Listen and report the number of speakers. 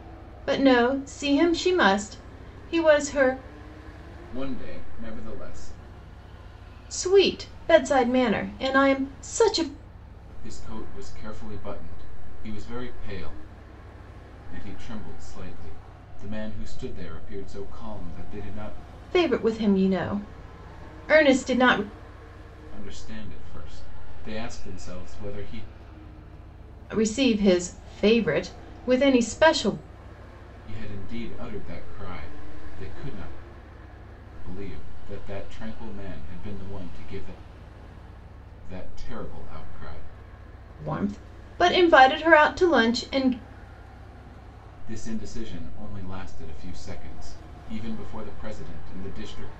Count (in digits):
2